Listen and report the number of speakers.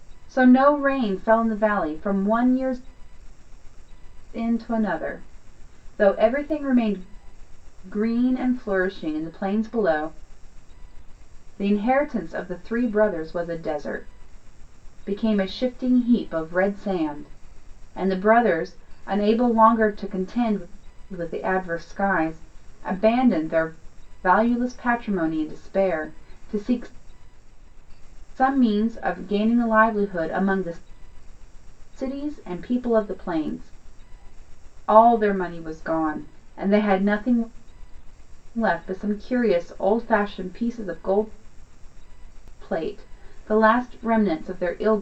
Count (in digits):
1